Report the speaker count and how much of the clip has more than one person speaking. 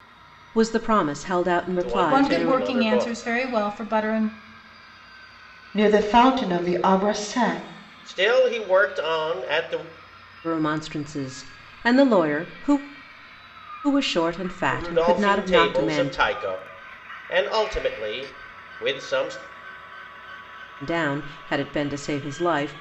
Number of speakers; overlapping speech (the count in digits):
4, about 13%